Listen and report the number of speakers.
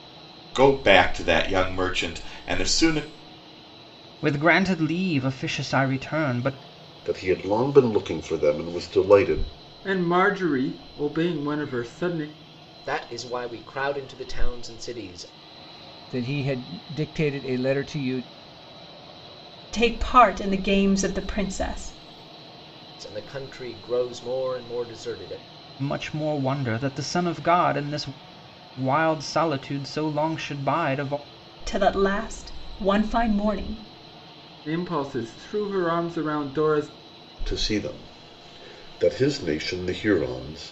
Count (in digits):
7